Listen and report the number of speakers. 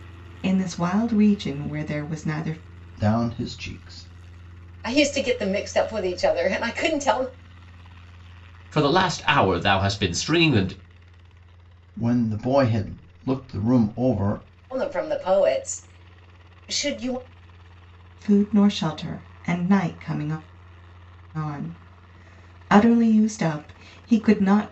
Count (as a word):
four